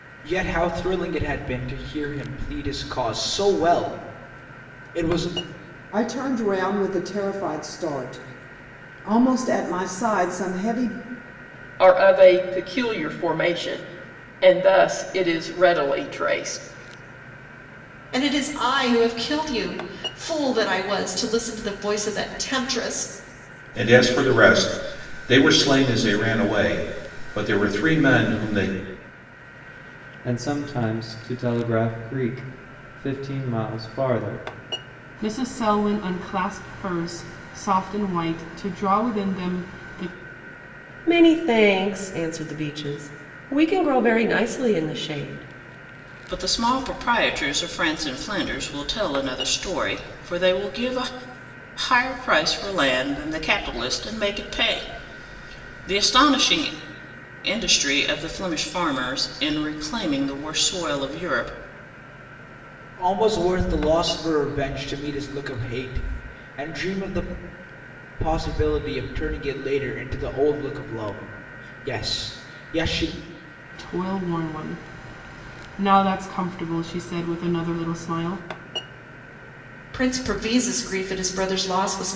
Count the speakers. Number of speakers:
nine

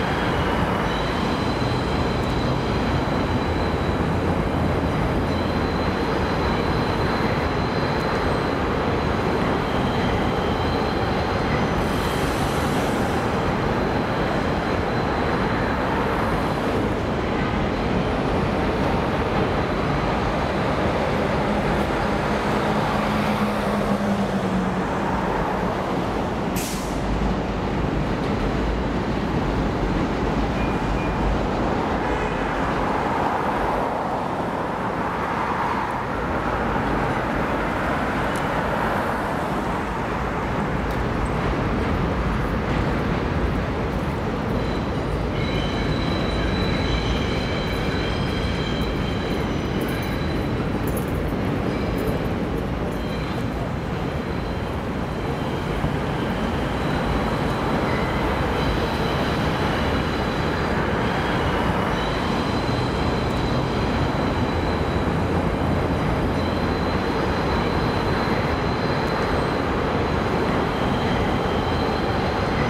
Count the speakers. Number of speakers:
zero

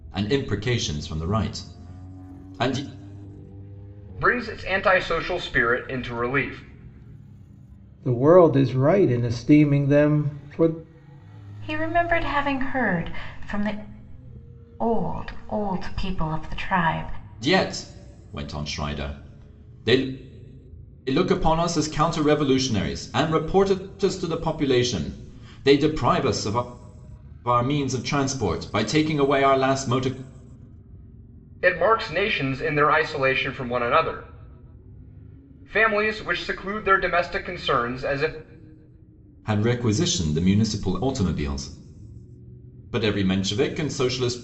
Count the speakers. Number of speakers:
four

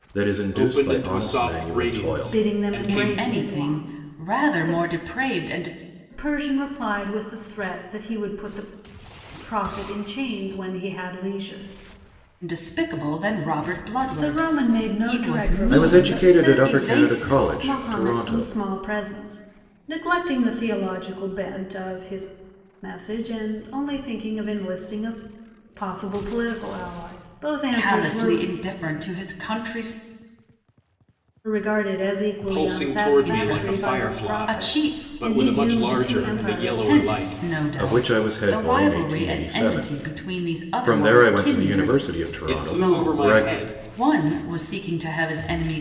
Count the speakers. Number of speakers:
four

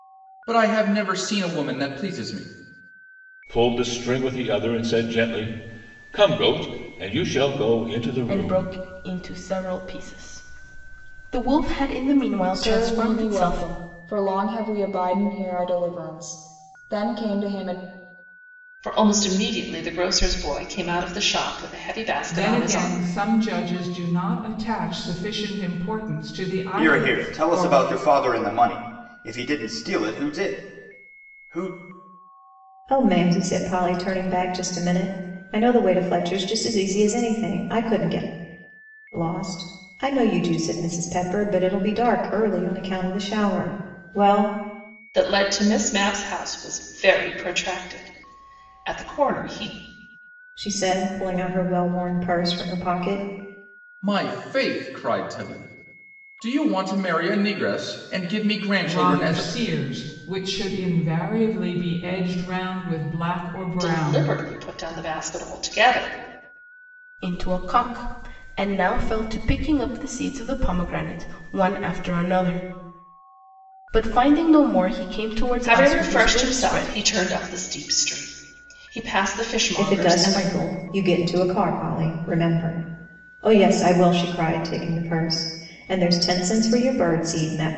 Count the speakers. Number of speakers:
eight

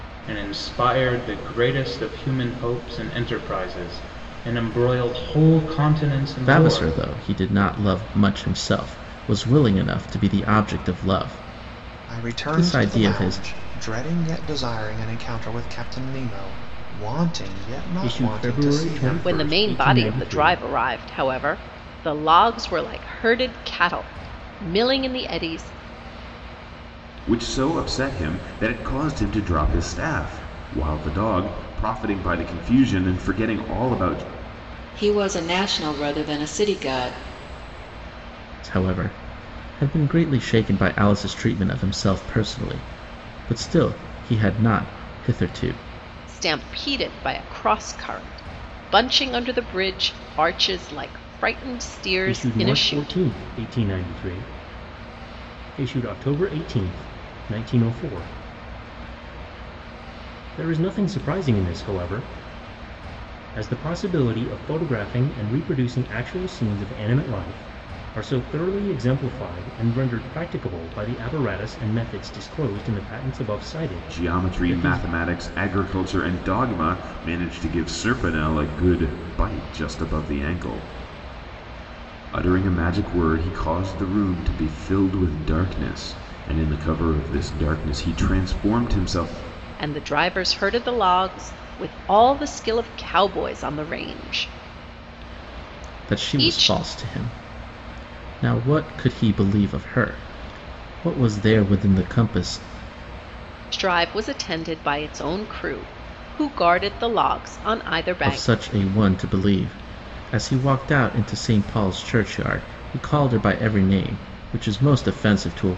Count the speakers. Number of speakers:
seven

